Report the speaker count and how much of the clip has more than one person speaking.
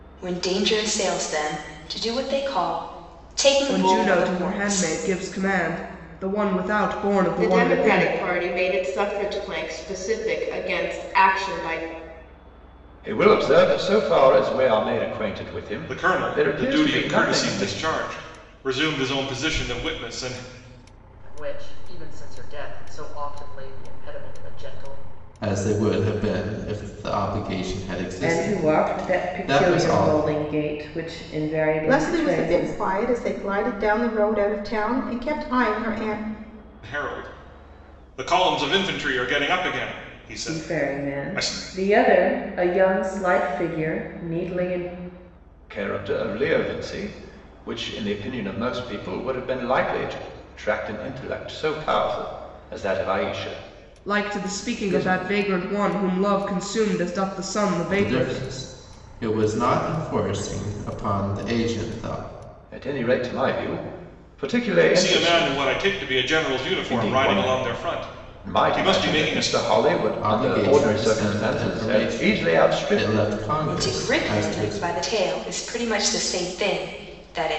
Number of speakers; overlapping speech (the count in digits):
9, about 23%